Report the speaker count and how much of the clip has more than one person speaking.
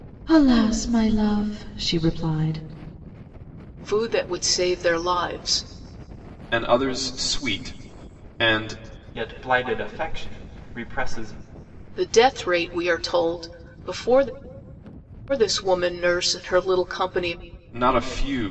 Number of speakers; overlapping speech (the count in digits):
4, no overlap